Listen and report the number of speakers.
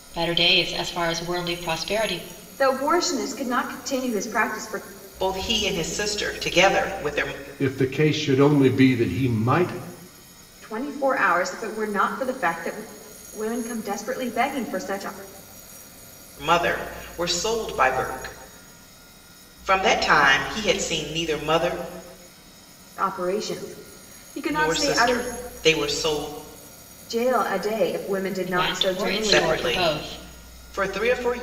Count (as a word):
four